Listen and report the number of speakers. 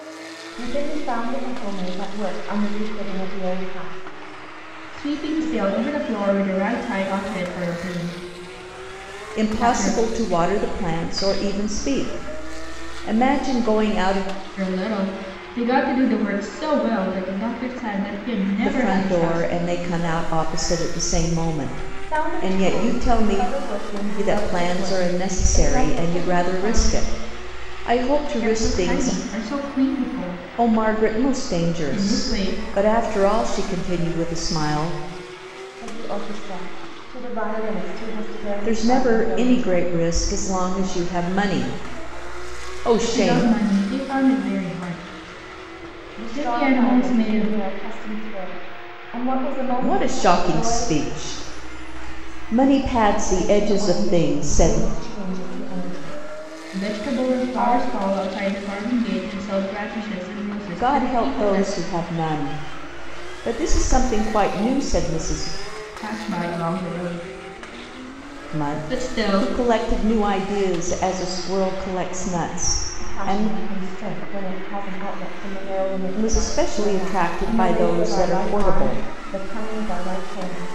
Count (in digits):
3